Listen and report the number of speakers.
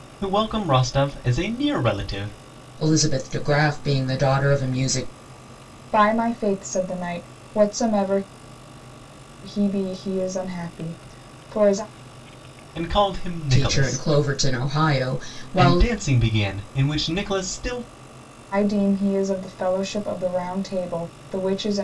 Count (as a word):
three